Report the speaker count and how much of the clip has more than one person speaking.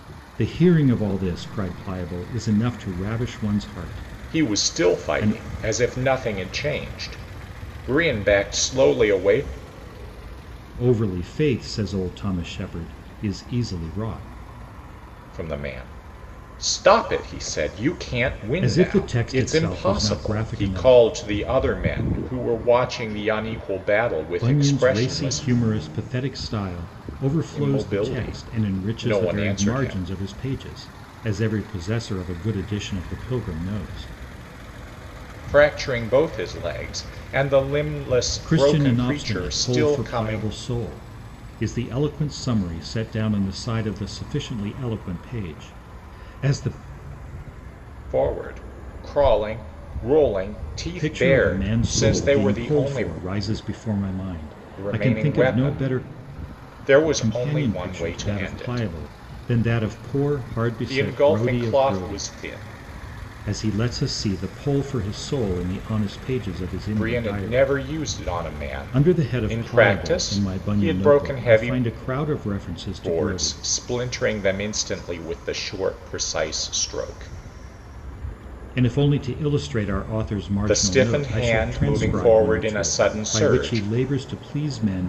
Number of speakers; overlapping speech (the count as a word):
two, about 28%